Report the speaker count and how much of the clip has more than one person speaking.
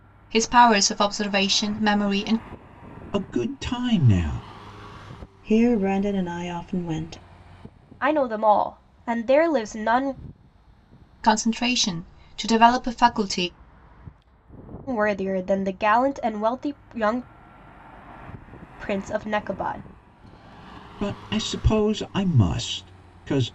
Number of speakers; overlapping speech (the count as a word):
four, no overlap